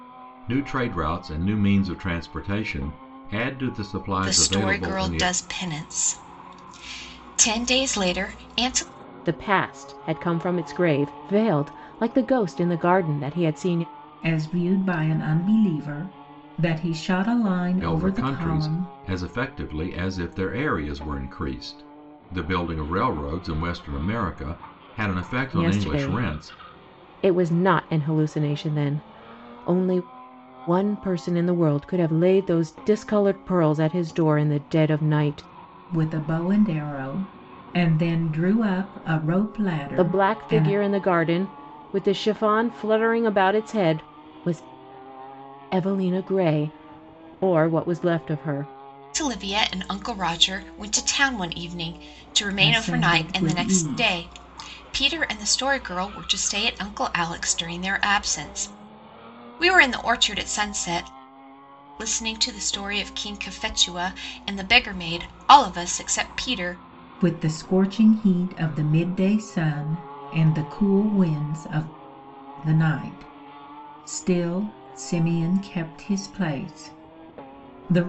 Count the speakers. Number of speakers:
four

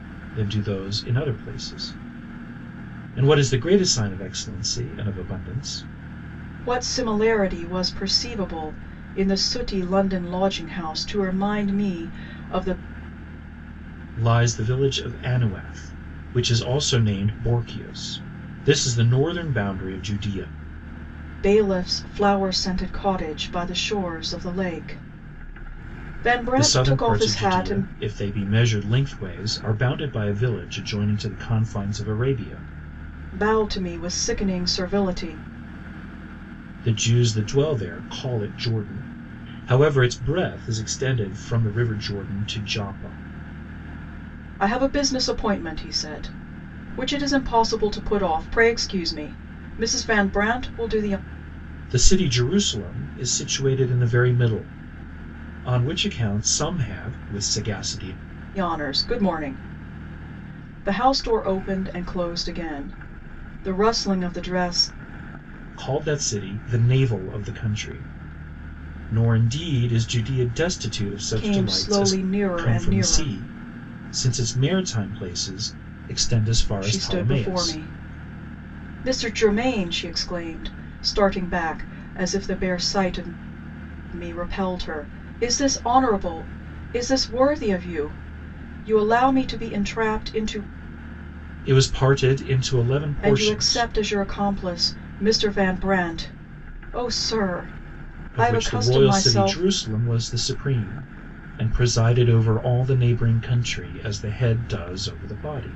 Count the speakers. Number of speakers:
two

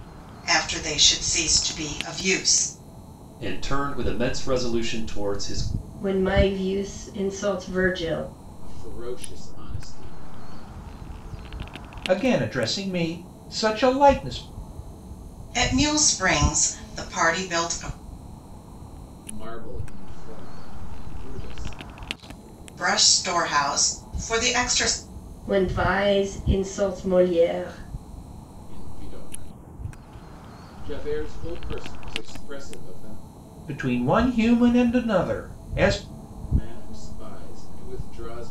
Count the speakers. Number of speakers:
five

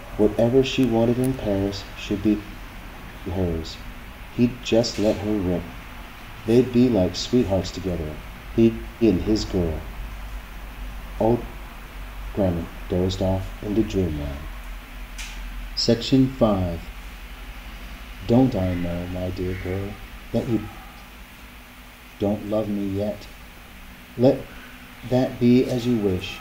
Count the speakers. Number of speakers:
one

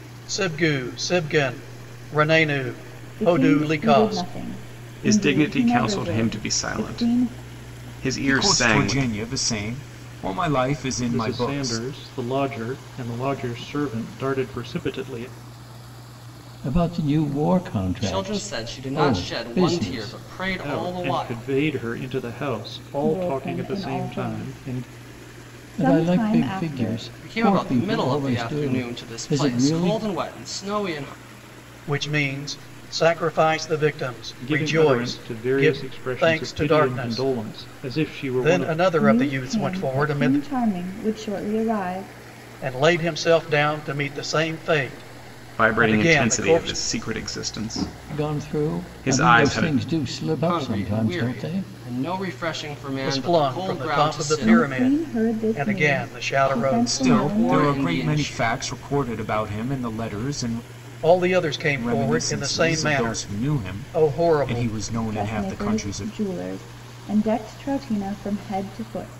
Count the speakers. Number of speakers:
seven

